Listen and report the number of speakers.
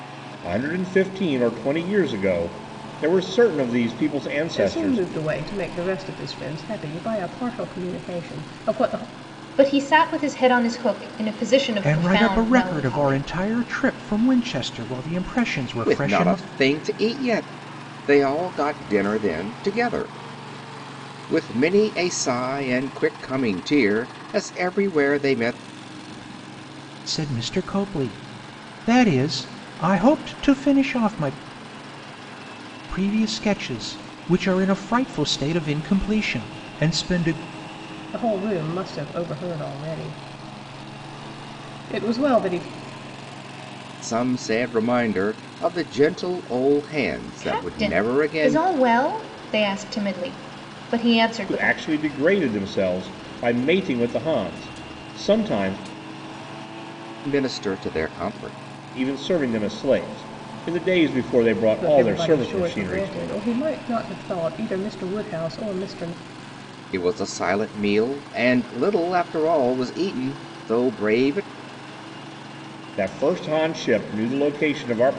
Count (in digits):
5